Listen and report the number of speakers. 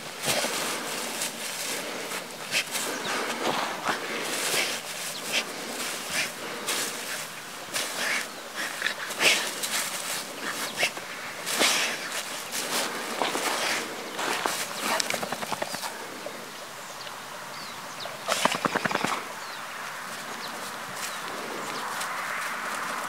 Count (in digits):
0